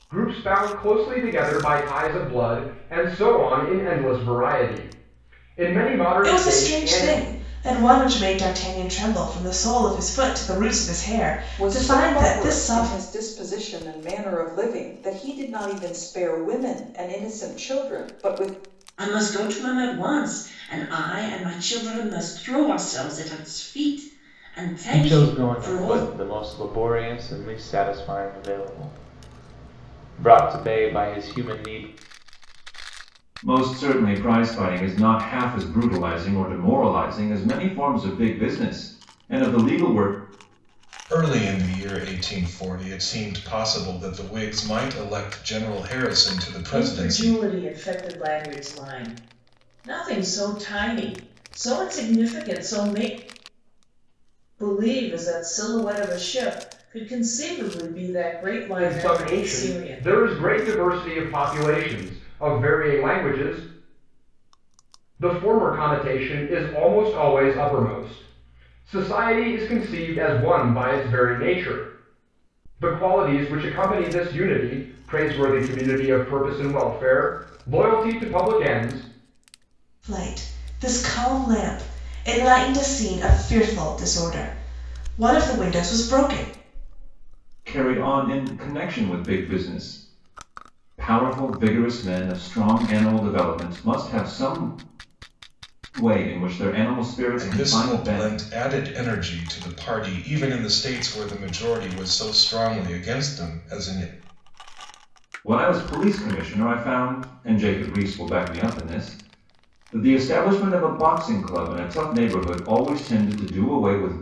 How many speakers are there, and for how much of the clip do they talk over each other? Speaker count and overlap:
8, about 6%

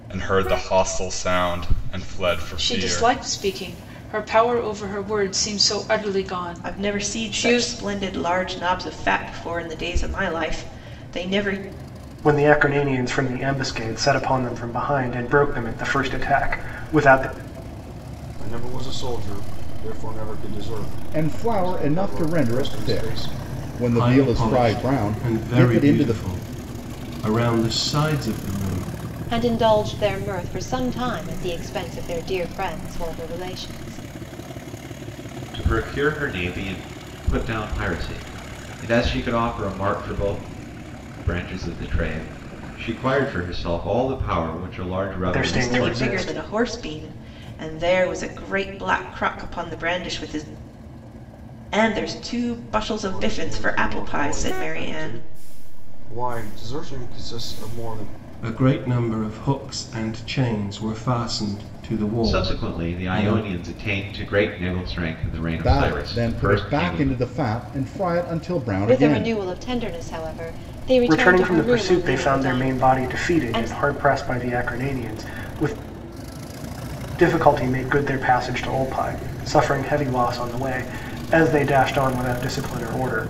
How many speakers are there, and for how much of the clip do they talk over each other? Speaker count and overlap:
9, about 19%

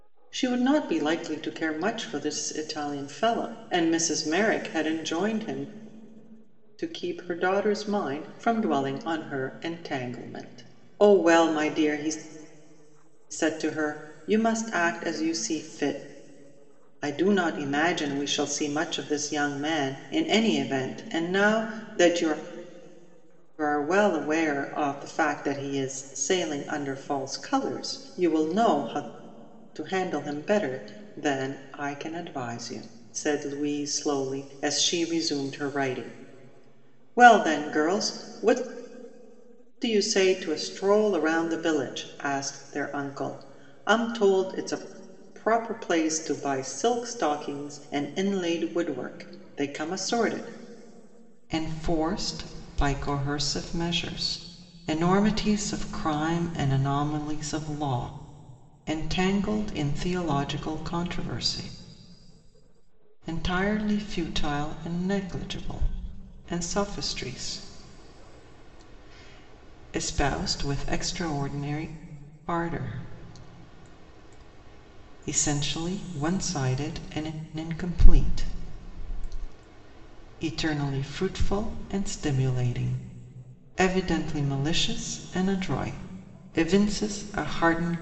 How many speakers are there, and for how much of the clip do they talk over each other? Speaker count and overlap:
1, no overlap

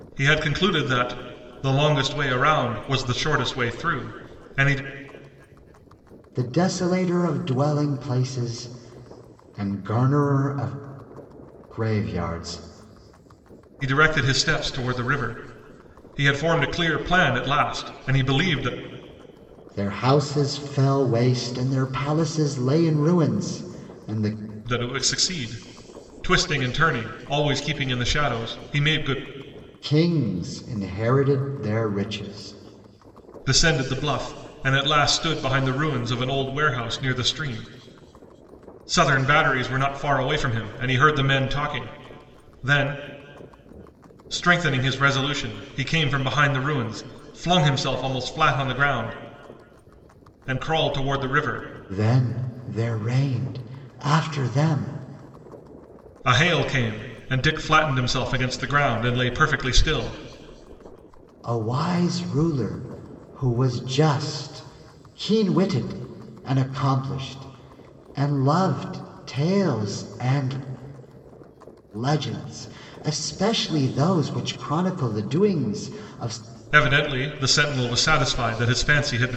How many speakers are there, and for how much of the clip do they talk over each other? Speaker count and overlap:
2, no overlap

